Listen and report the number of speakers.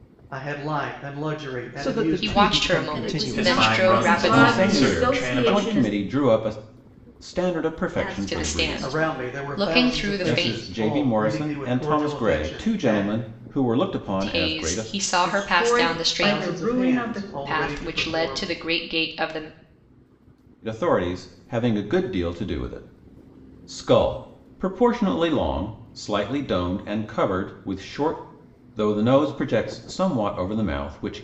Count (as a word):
seven